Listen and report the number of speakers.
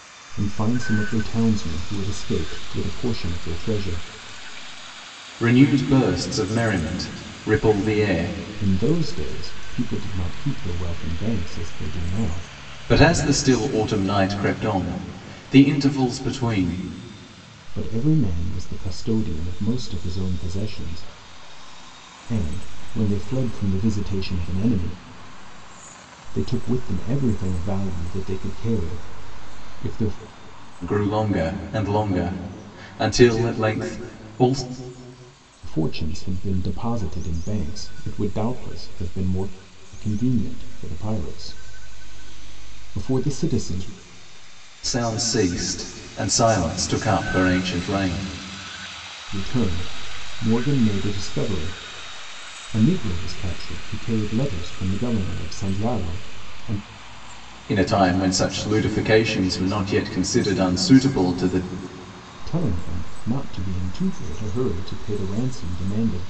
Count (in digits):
2